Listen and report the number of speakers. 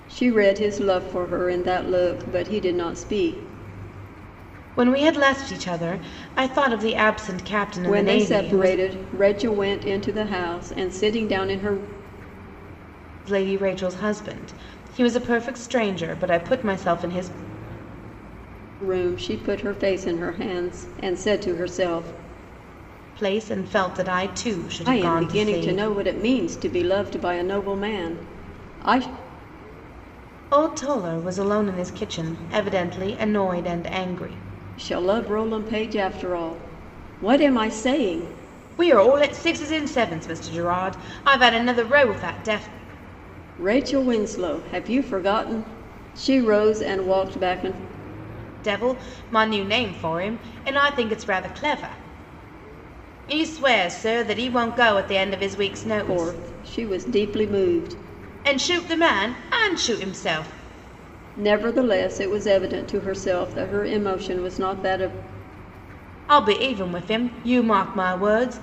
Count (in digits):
2